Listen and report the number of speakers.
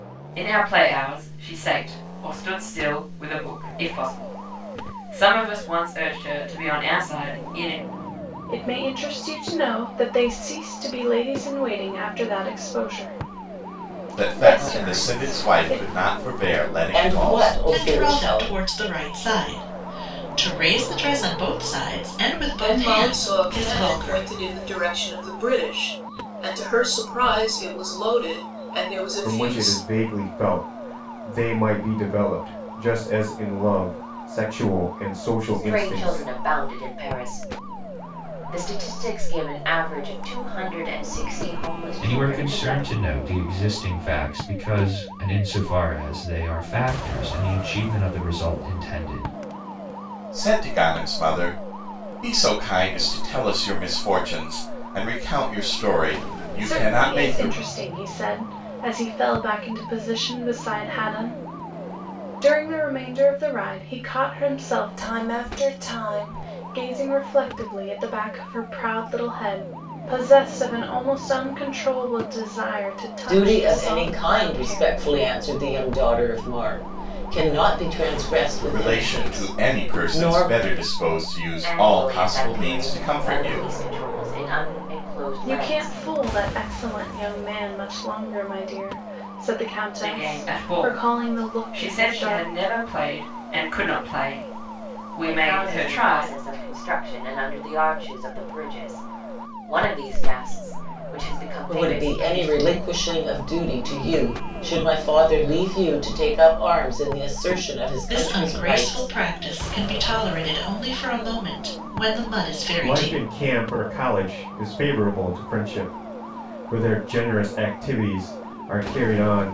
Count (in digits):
9